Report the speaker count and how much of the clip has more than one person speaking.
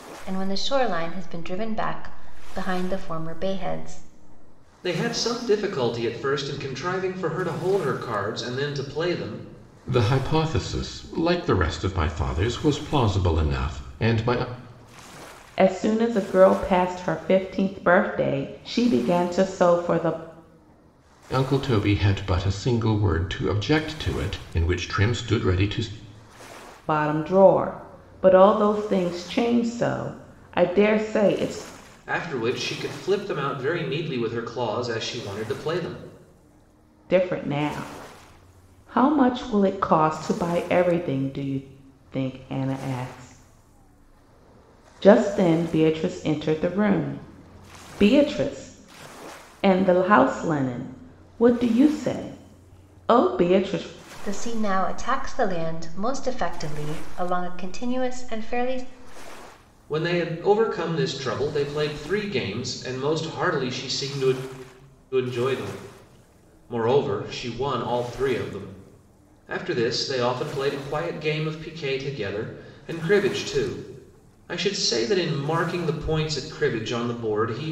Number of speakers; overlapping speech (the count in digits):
4, no overlap